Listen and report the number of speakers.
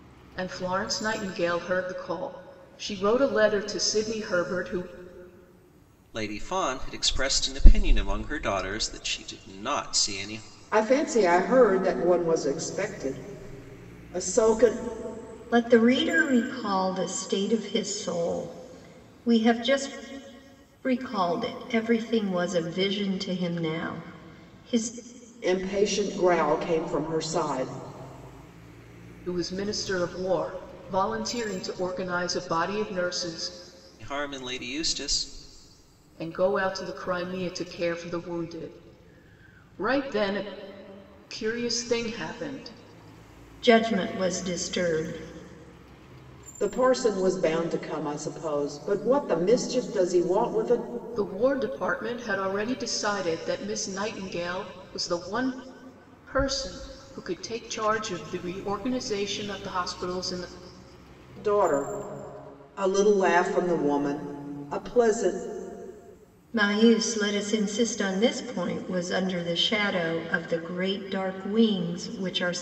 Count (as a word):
four